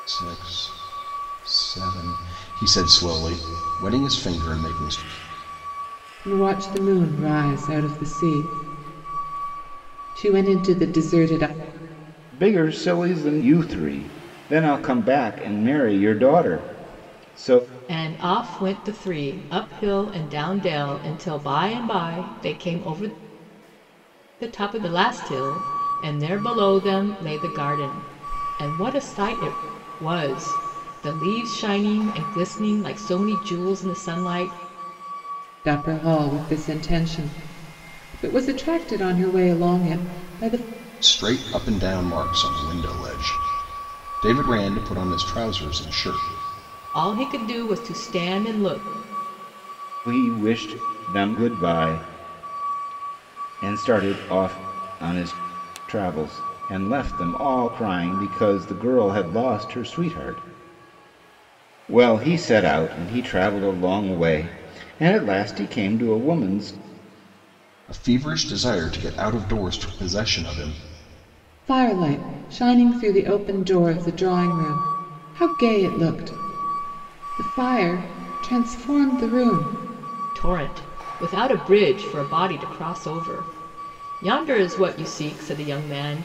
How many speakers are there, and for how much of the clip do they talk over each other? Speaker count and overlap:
4, no overlap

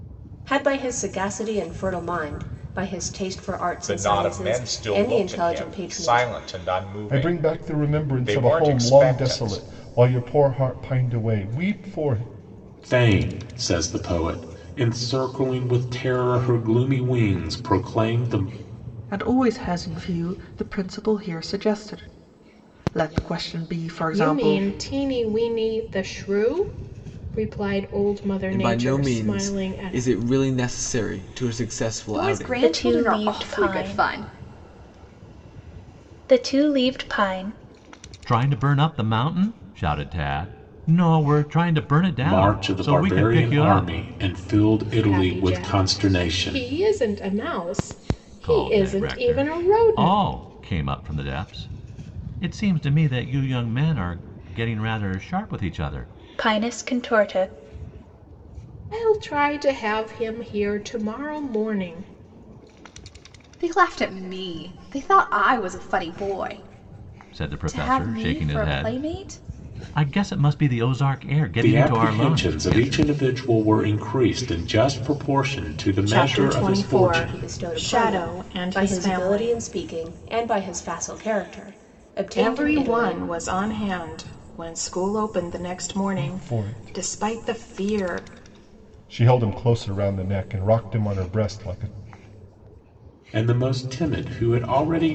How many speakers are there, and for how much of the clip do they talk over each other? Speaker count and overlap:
10, about 26%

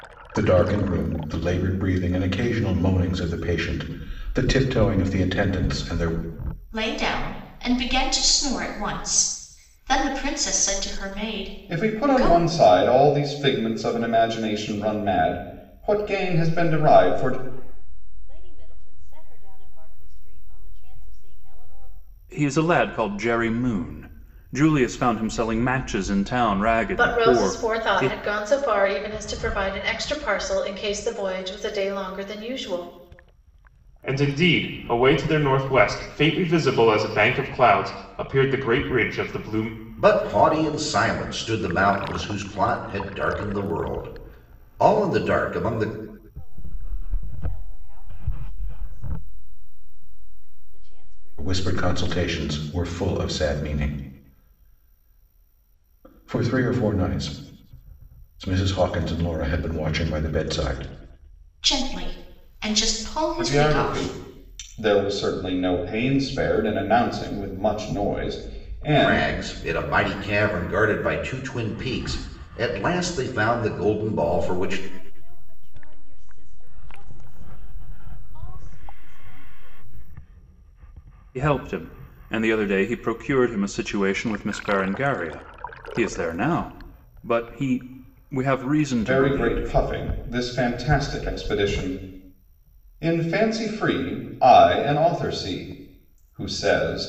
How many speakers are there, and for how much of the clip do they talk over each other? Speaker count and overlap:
8, about 7%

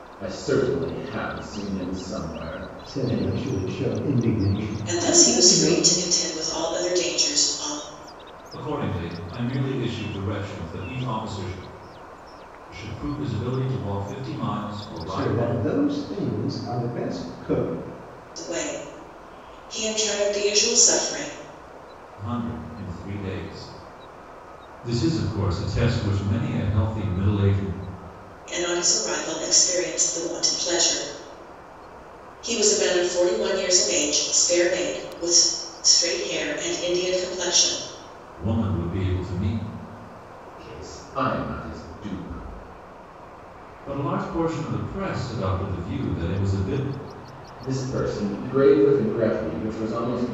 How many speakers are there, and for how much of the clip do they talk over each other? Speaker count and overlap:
4, about 4%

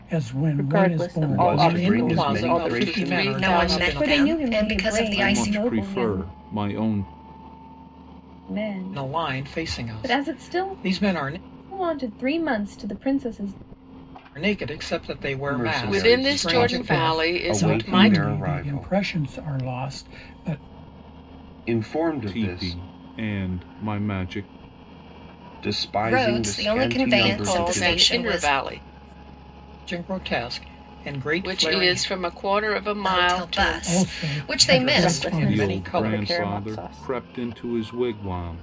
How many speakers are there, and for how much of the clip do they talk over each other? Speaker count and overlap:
8, about 49%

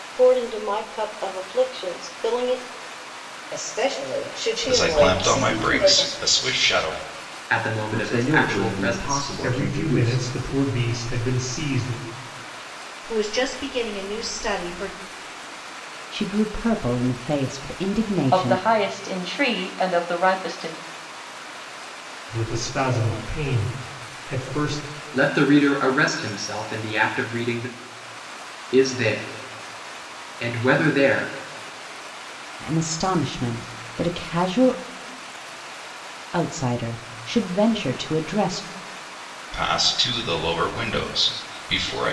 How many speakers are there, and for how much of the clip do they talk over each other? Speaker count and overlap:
9, about 10%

